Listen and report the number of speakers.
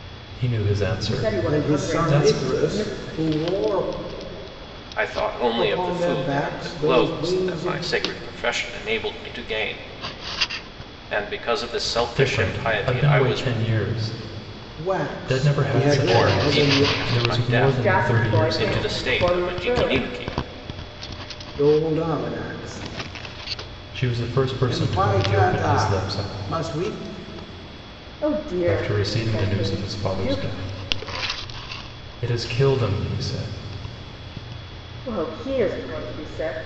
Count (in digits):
4